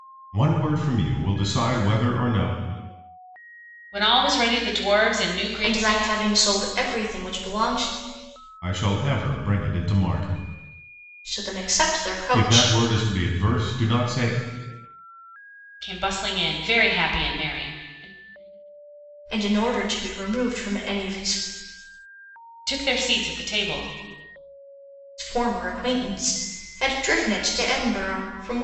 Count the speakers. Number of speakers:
3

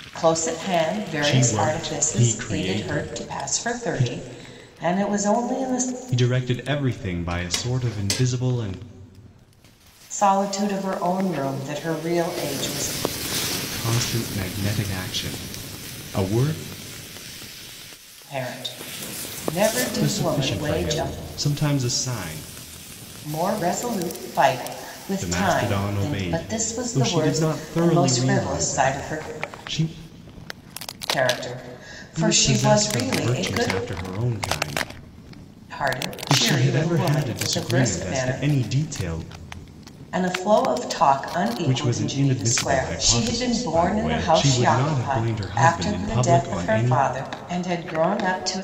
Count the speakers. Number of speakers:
2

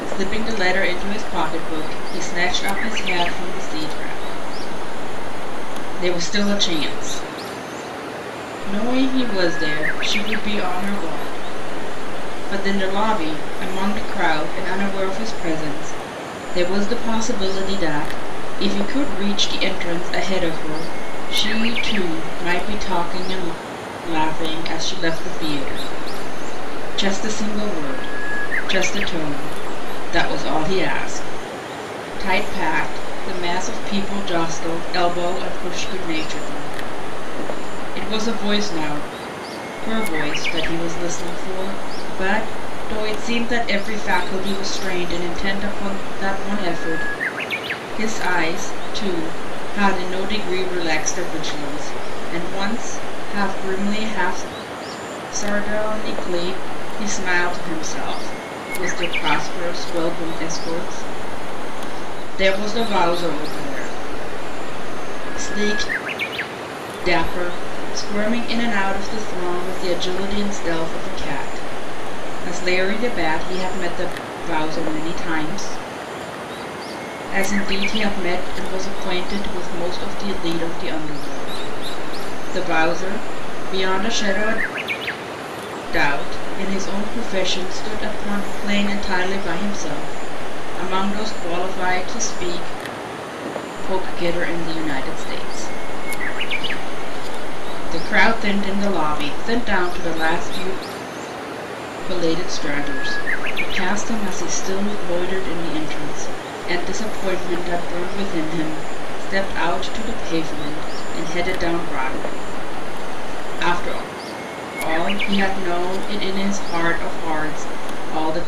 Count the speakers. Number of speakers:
1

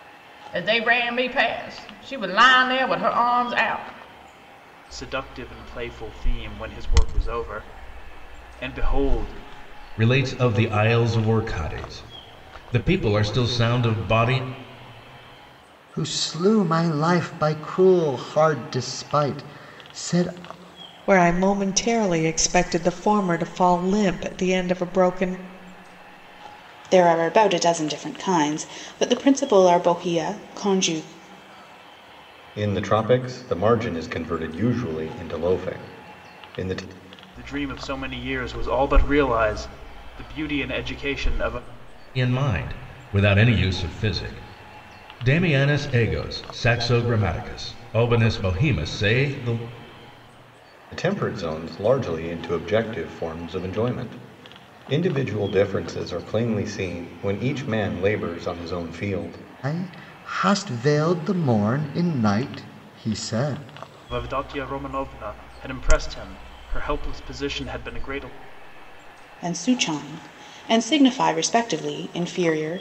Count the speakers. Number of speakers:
7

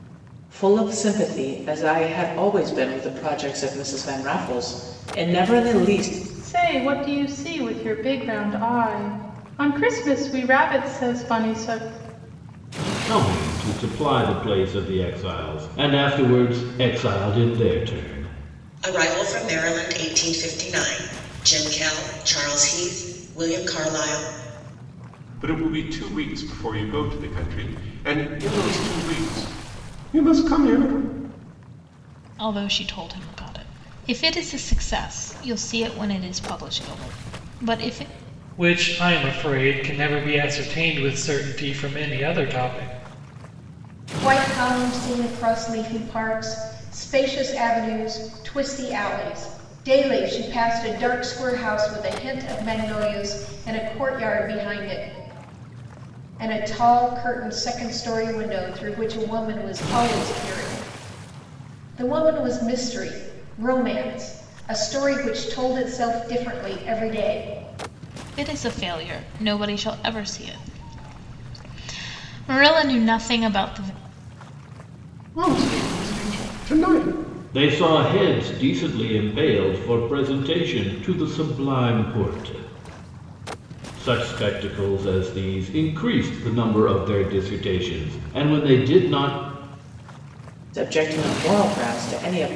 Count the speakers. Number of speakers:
8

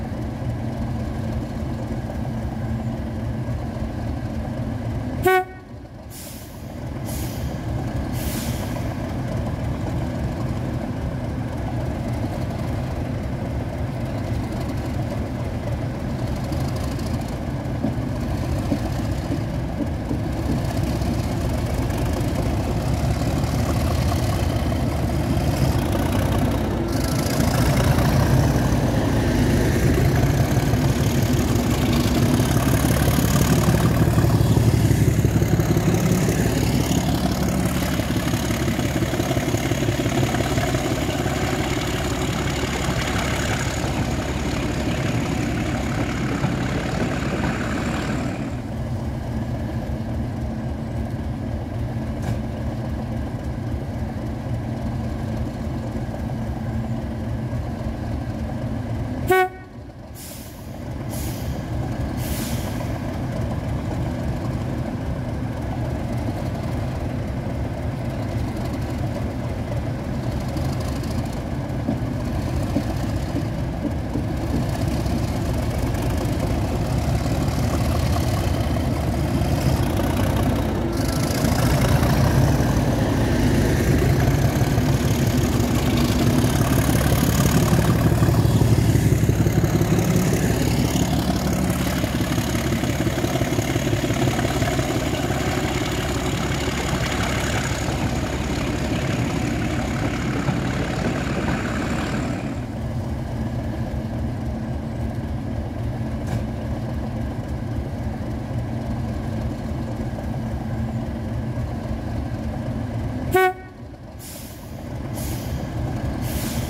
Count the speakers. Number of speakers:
0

